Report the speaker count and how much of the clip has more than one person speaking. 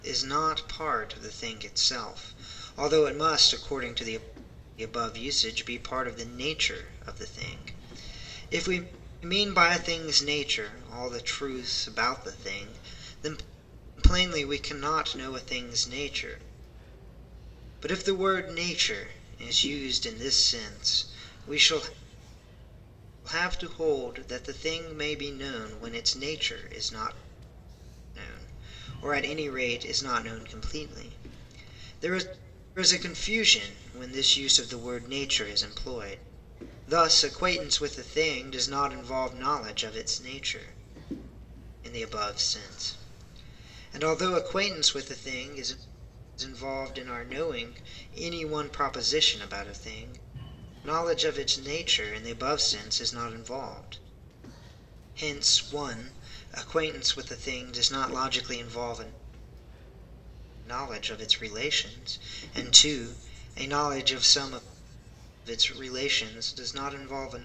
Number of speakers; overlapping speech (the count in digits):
1, no overlap